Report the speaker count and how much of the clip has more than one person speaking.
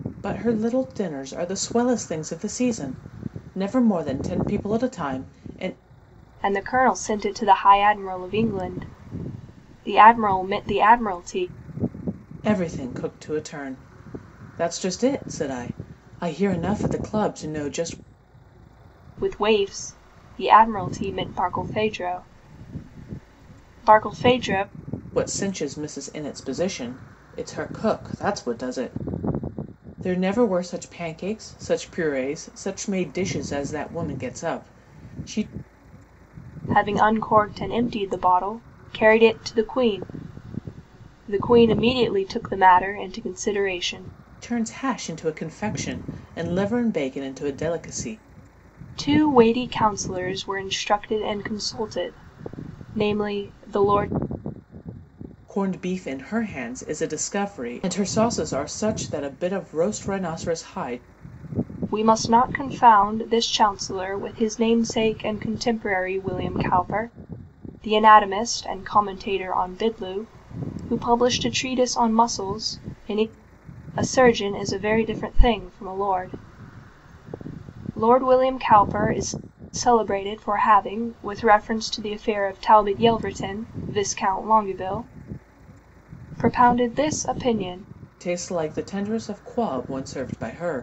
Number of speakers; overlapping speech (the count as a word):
two, no overlap